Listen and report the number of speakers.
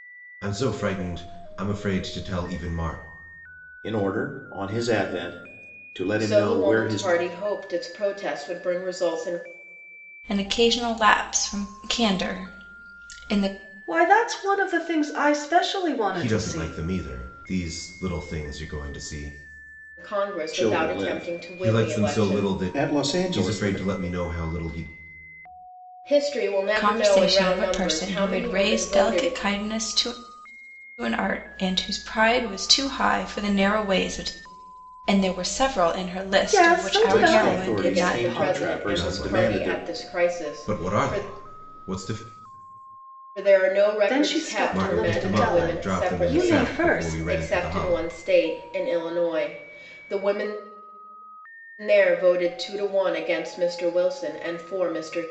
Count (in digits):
5